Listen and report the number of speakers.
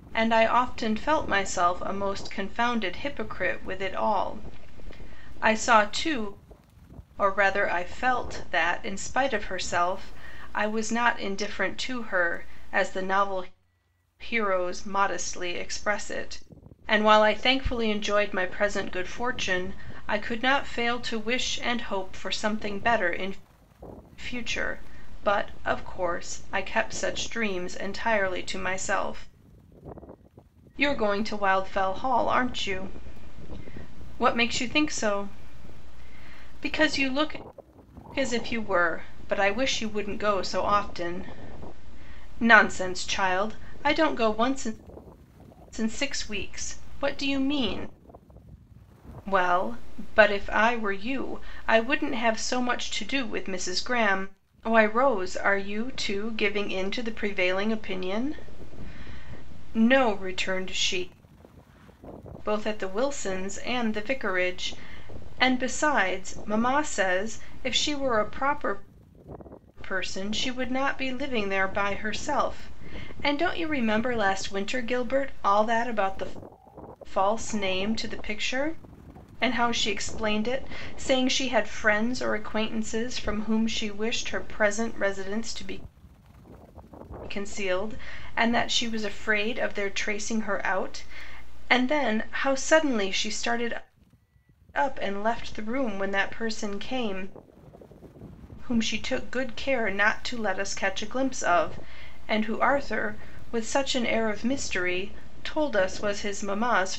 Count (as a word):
one